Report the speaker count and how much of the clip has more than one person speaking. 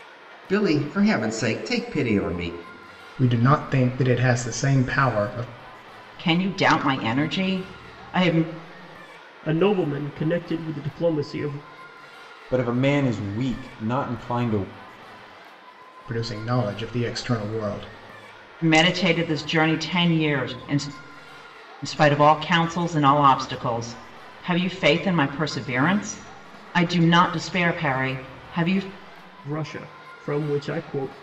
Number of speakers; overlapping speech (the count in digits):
5, no overlap